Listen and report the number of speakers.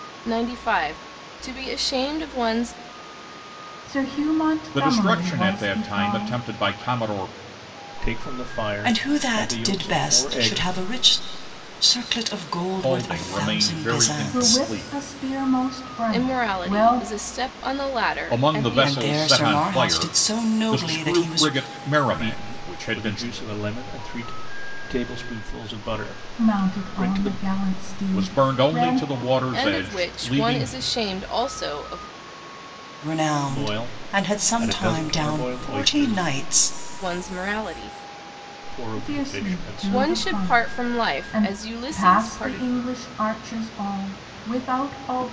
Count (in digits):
5